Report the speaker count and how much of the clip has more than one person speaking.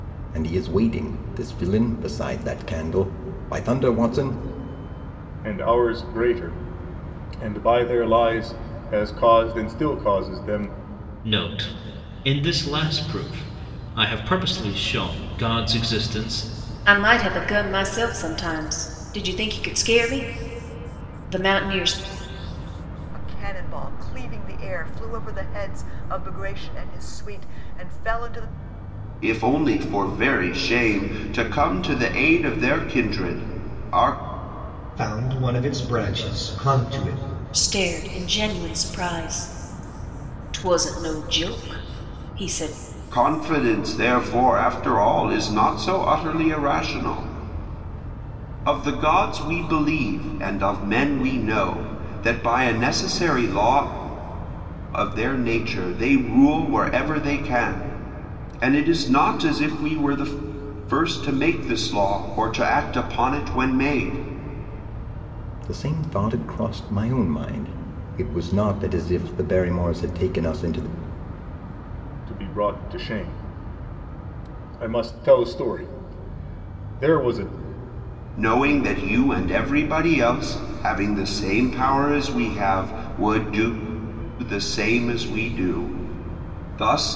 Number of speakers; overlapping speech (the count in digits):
7, no overlap